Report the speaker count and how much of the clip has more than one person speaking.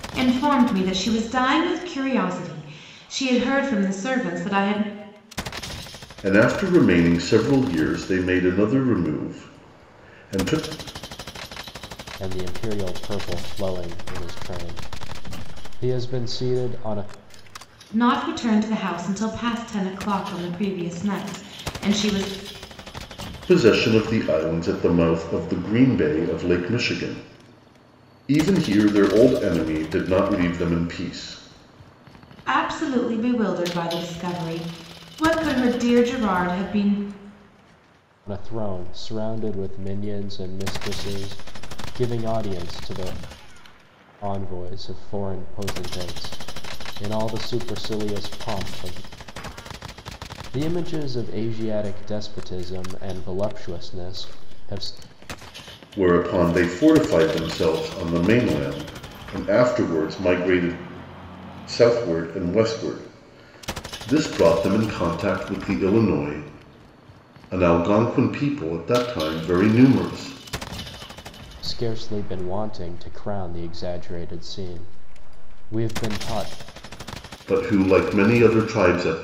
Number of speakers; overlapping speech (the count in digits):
3, no overlap